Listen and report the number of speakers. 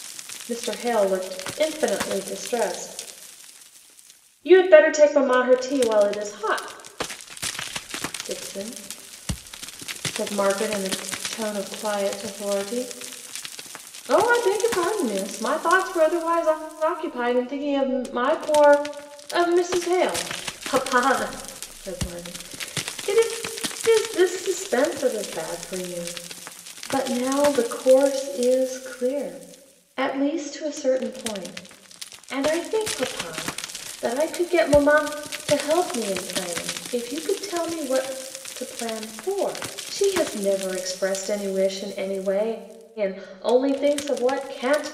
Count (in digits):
1